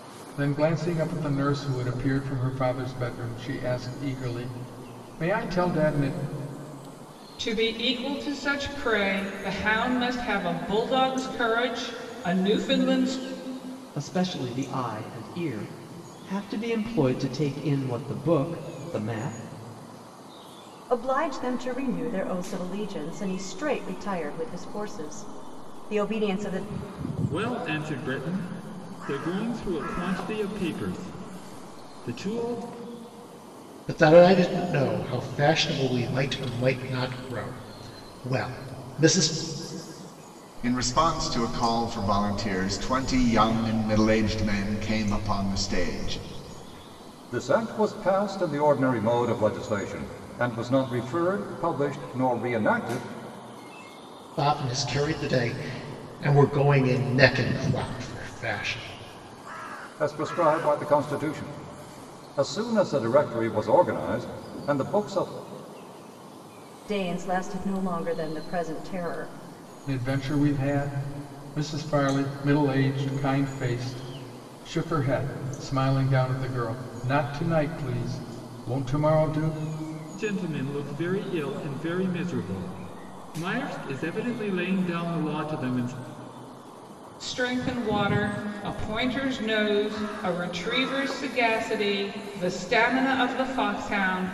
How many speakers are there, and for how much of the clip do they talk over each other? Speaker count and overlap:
8, no overlap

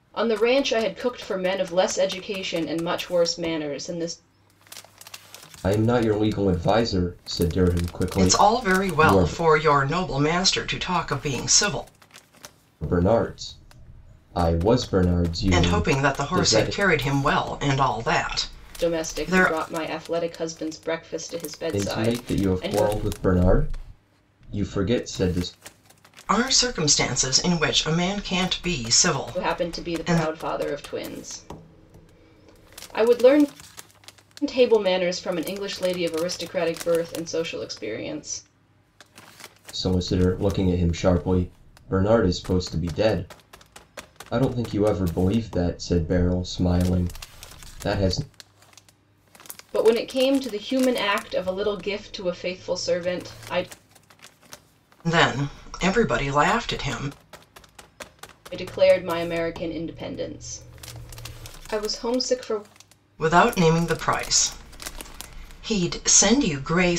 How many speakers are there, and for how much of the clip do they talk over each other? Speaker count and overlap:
3, about 8%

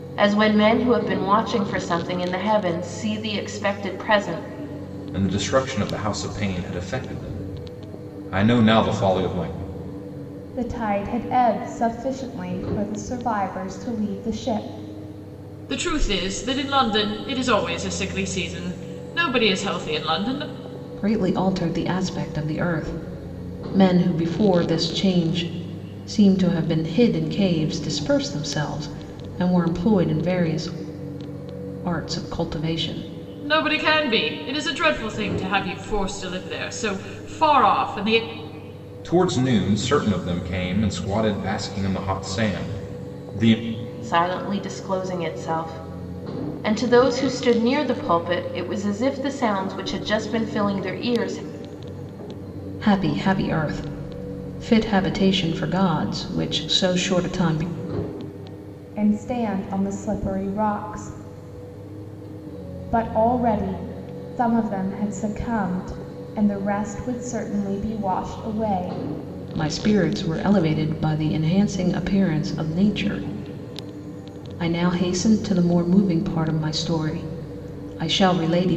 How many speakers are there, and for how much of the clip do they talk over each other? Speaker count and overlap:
5, no overlap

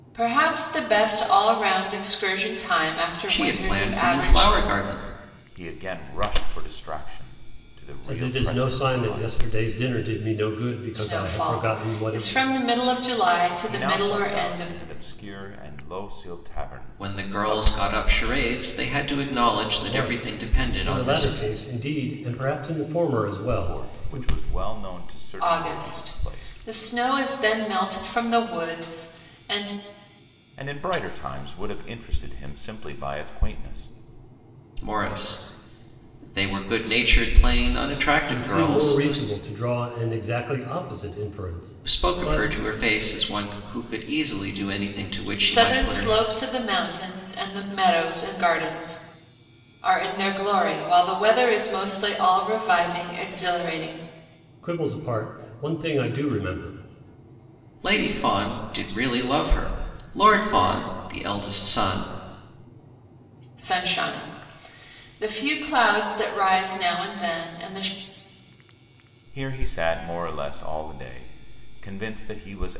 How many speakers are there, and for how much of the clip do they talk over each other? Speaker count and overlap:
4, about 16%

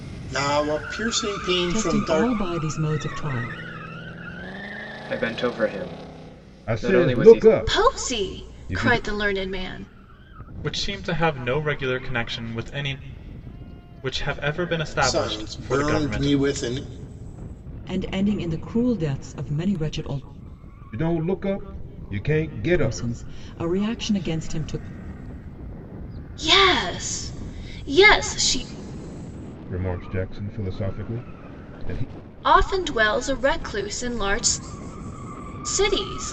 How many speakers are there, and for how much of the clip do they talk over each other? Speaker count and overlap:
6, about 13%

